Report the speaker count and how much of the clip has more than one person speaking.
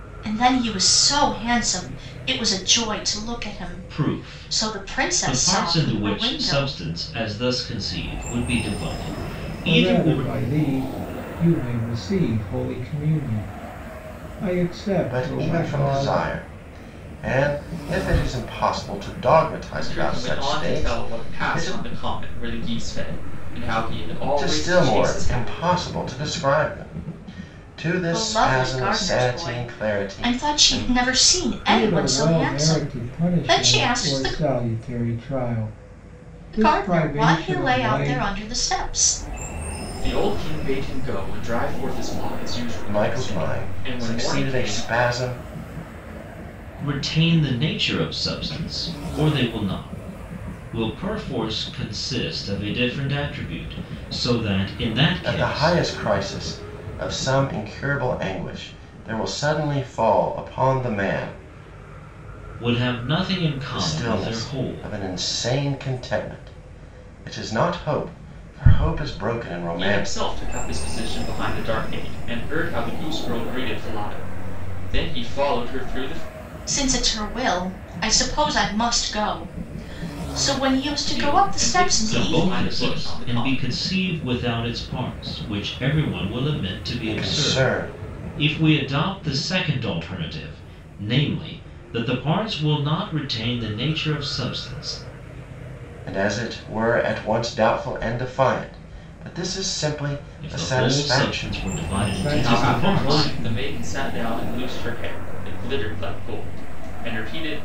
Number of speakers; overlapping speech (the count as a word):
five, about 25%